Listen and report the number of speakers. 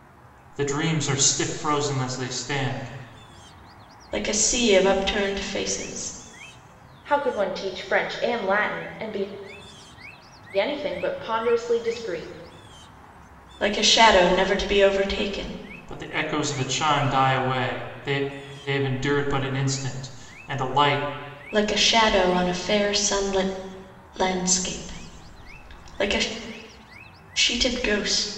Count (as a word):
three